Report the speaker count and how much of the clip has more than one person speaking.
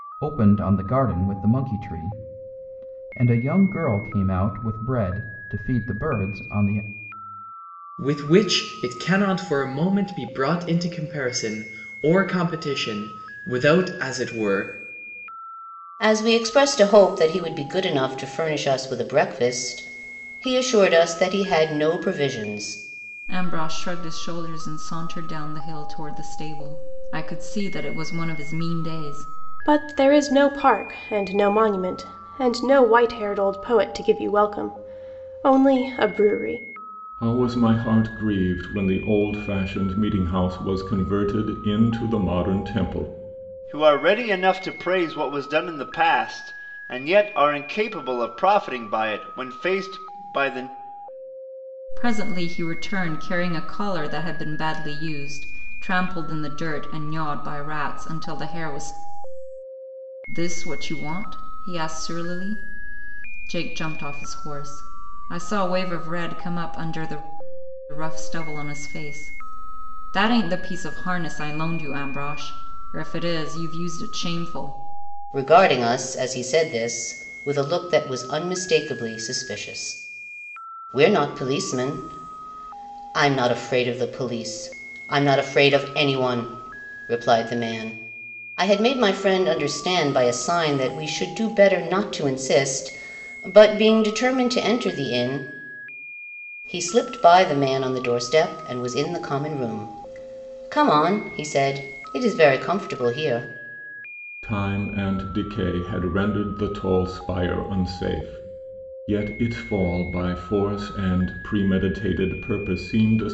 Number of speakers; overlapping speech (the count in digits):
7, no overlap